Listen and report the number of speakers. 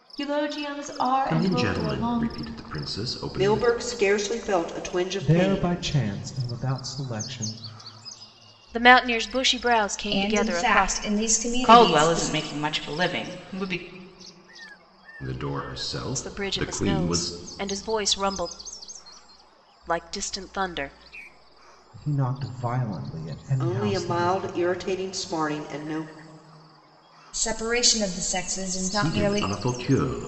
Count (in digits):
7